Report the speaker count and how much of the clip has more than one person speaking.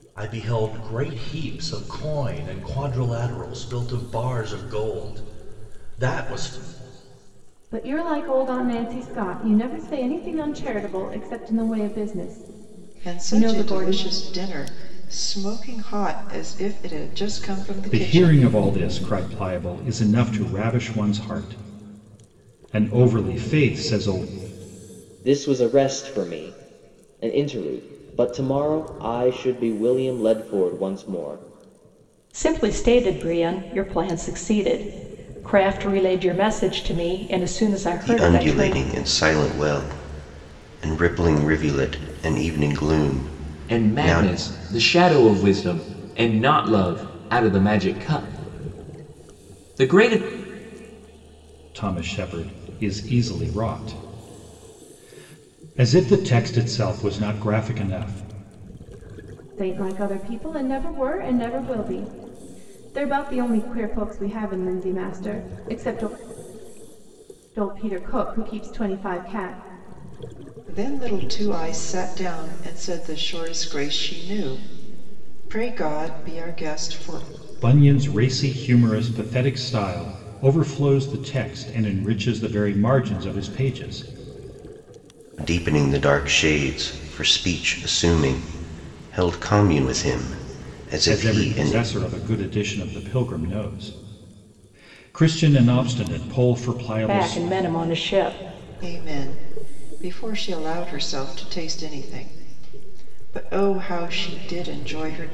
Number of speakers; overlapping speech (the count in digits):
8, about 4%